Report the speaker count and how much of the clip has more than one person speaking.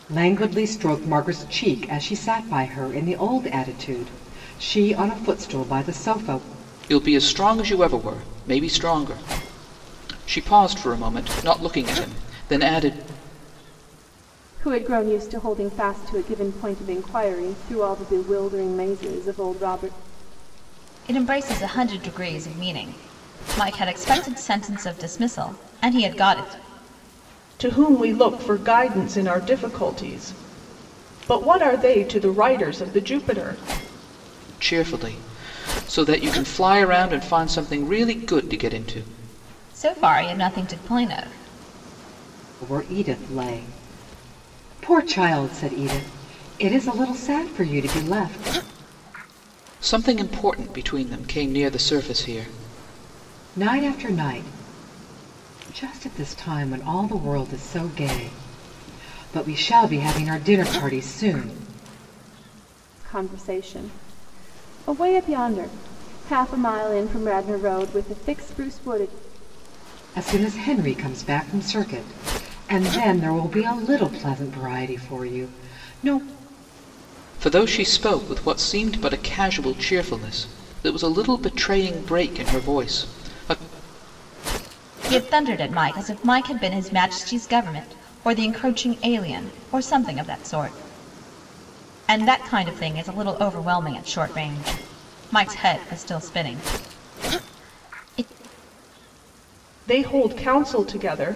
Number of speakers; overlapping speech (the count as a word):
five, no overlap